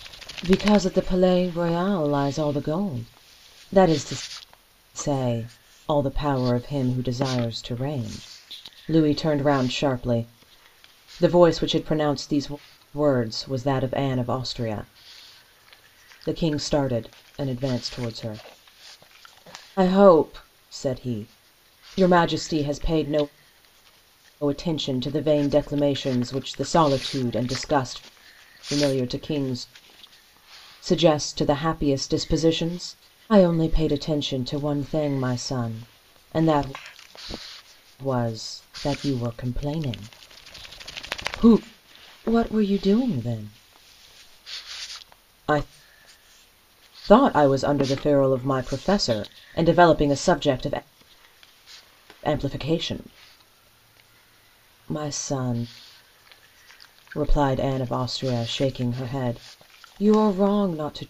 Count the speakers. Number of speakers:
1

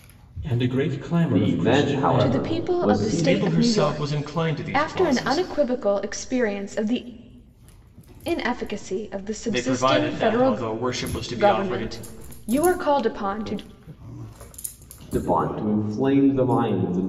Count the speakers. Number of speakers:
4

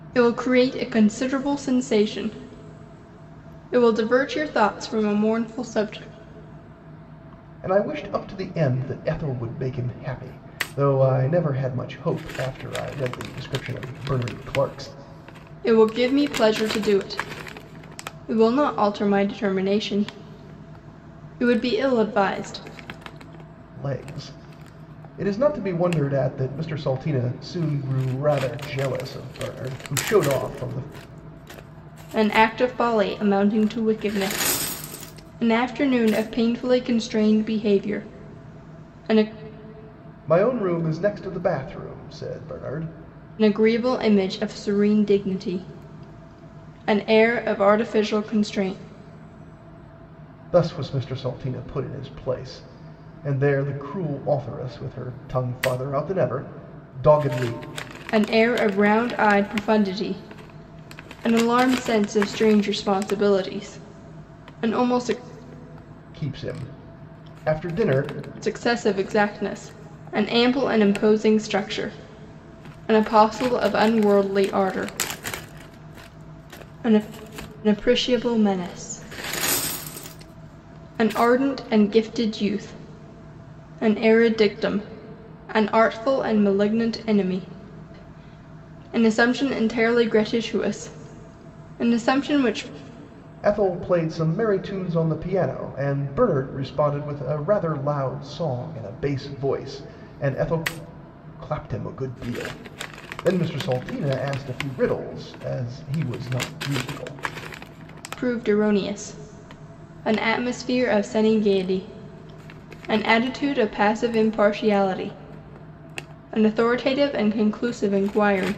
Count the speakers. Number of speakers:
2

